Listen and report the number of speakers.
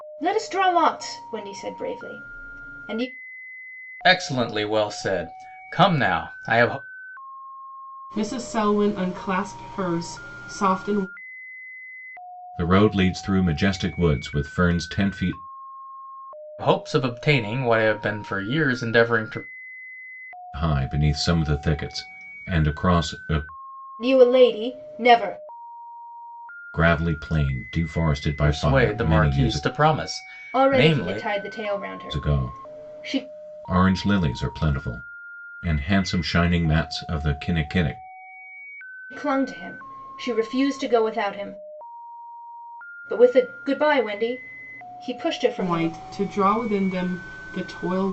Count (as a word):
four